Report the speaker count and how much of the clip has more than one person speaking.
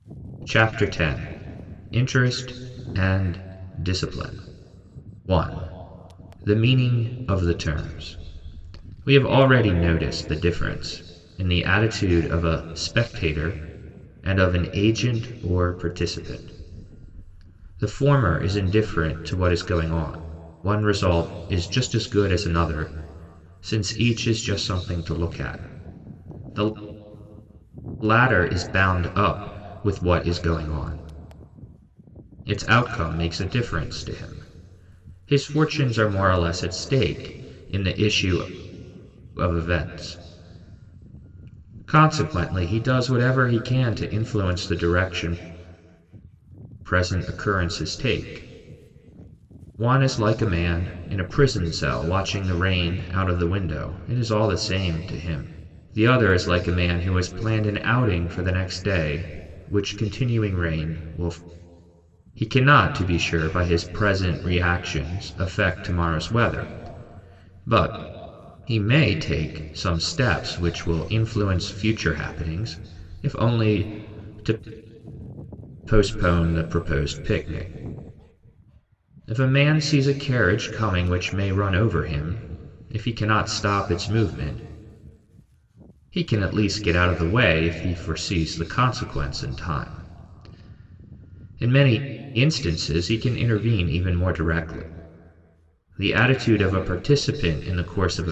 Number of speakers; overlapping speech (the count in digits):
1, no overlap